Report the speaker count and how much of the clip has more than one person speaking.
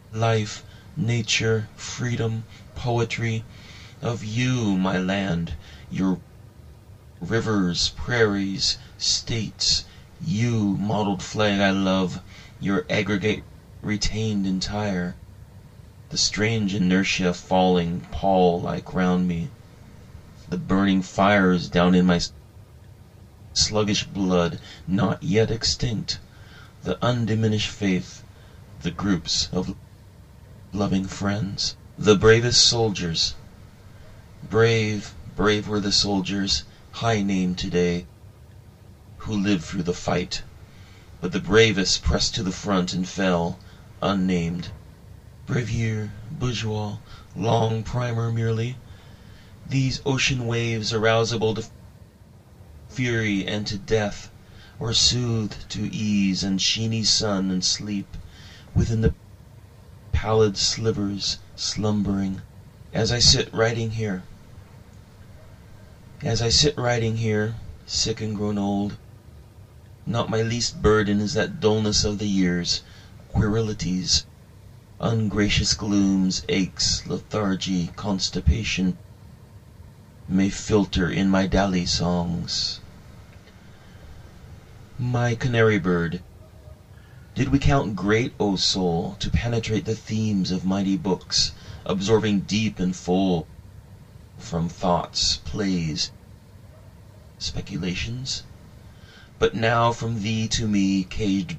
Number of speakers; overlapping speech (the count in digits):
1, no overlap